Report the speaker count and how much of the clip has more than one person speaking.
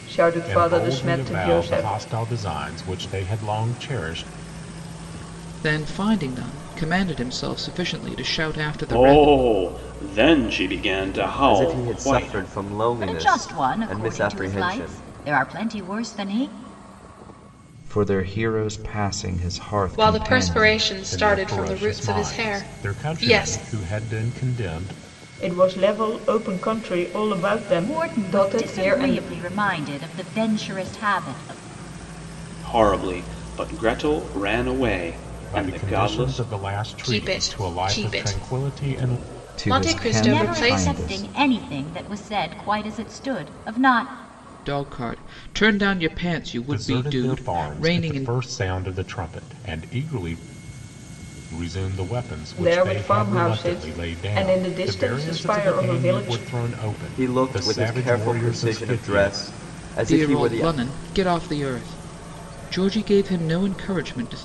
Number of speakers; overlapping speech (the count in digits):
8, about 37%